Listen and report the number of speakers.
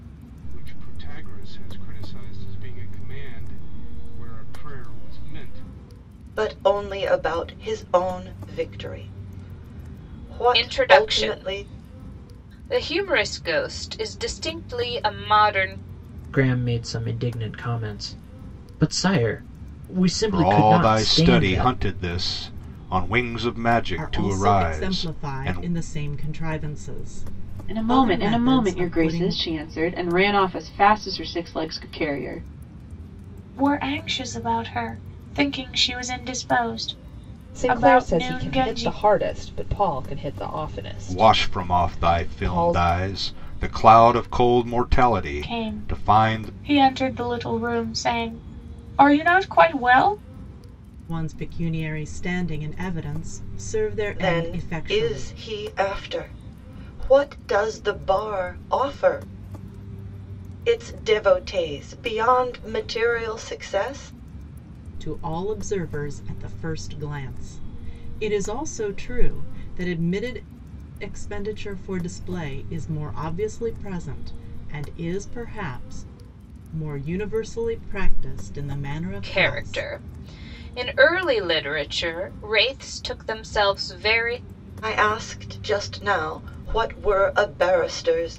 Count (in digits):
9